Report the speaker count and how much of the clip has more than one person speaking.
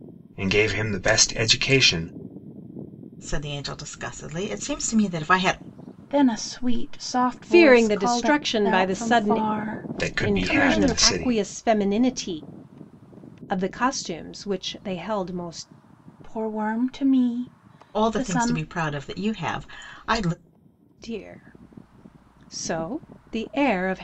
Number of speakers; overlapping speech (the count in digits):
4, about 16%